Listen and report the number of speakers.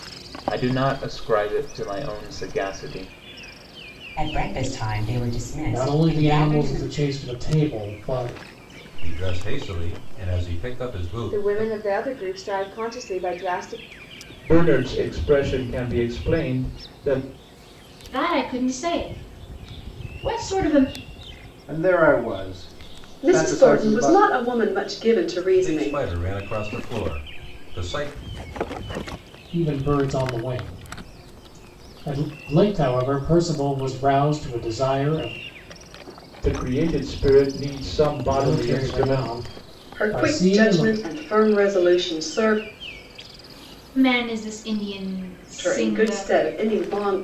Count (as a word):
nine